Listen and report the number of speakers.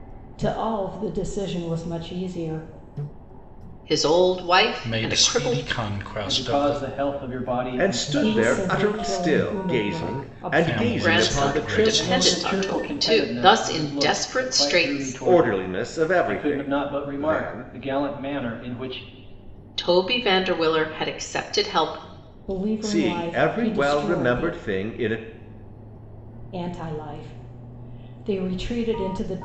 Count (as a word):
five